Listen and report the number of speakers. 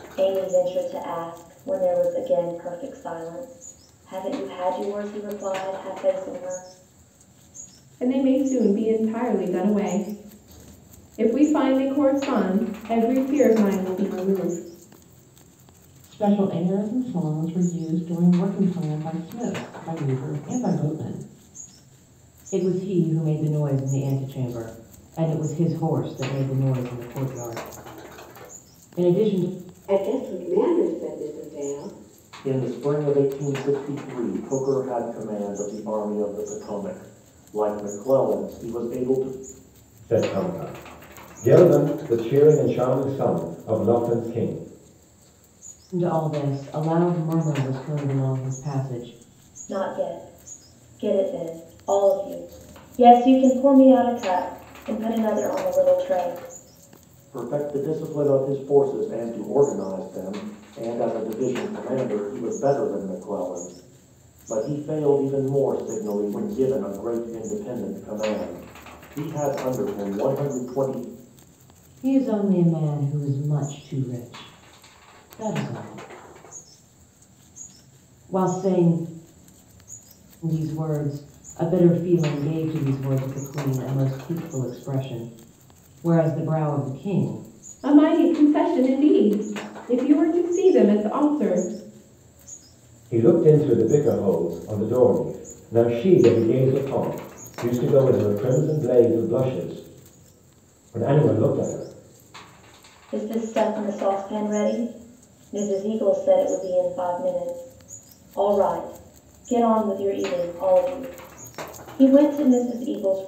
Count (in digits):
7